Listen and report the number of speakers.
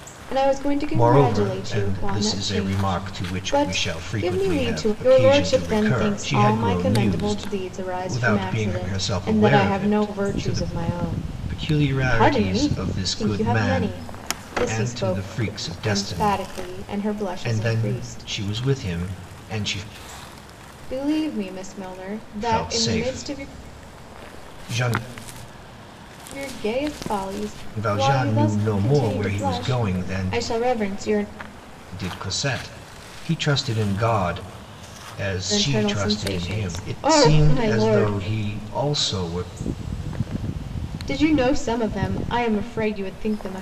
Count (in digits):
2